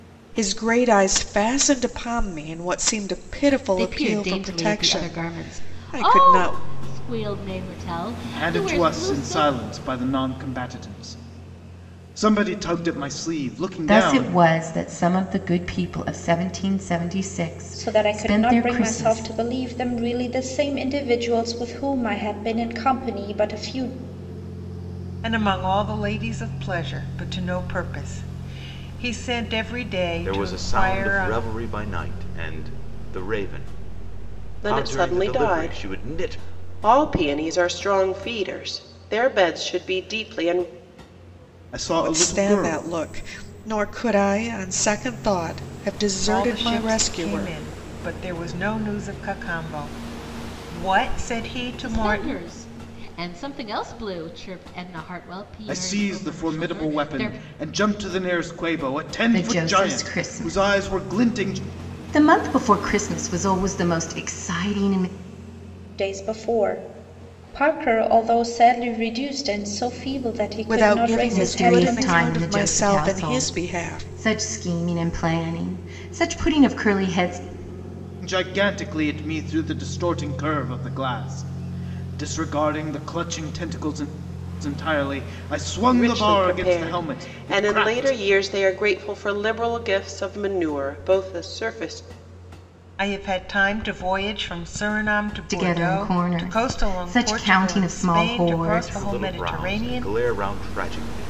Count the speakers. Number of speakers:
8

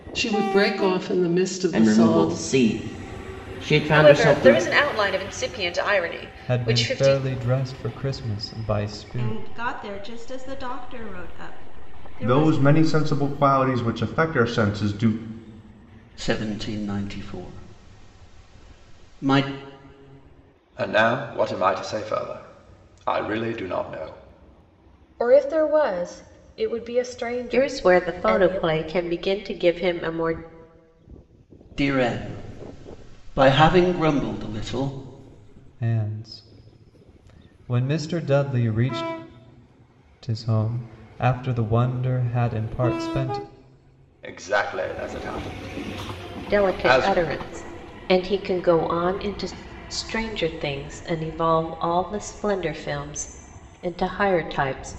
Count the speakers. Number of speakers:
10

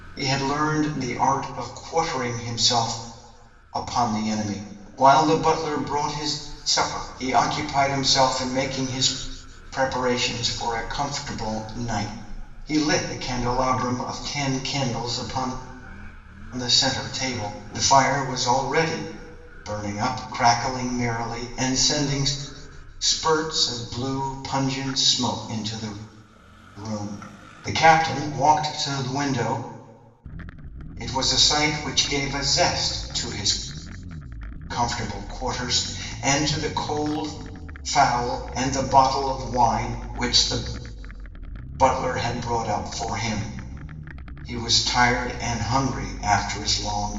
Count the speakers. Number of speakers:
1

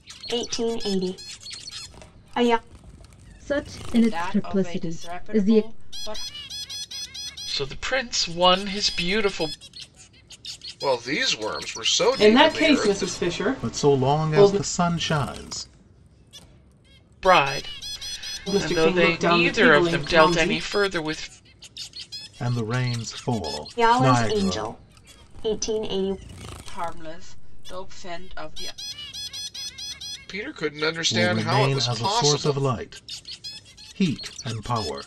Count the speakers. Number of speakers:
7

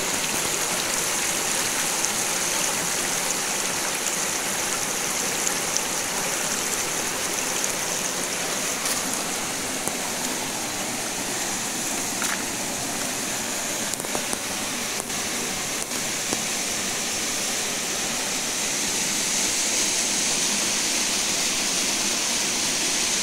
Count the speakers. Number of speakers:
0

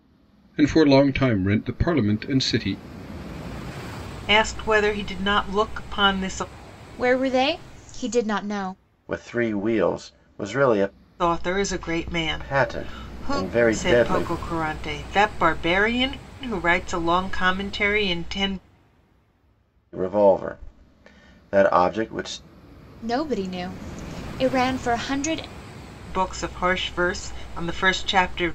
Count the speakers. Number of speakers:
4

